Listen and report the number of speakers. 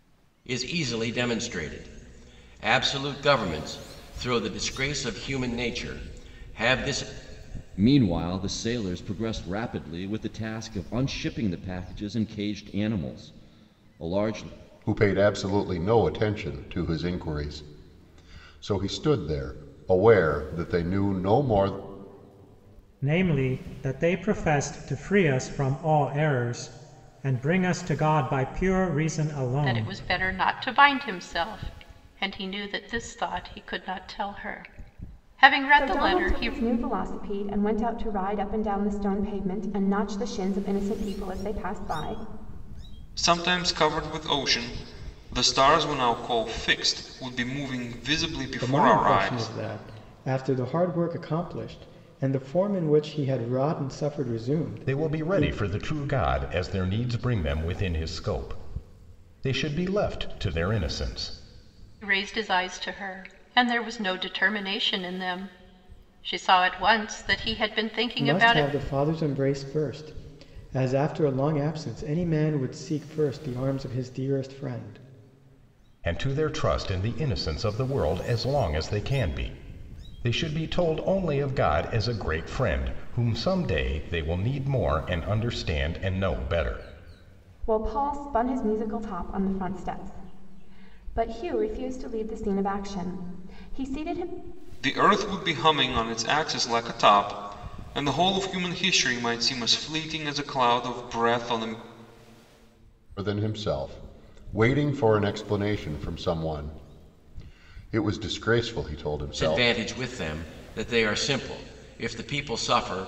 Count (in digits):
9